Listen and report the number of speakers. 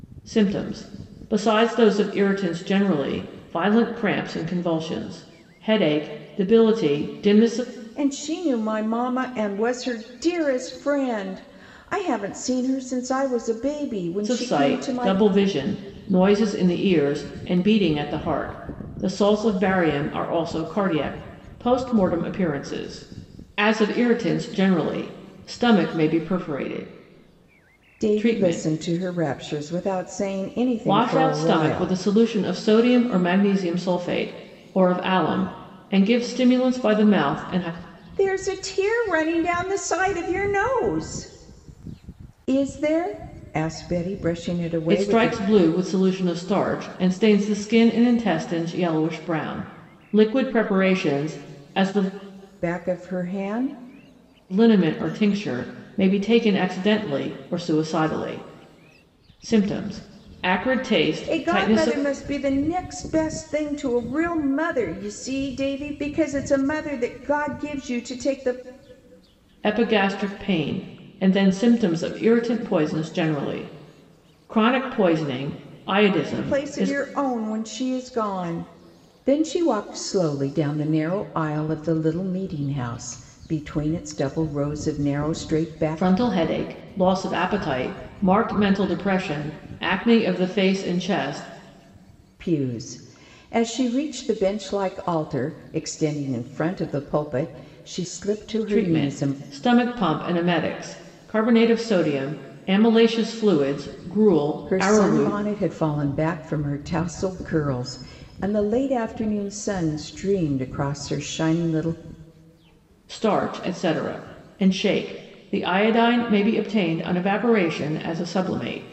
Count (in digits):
2